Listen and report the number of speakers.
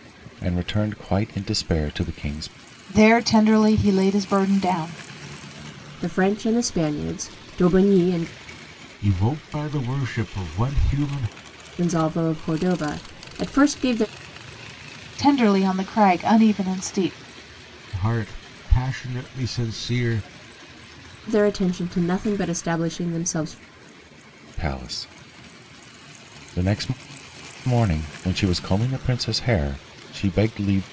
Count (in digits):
4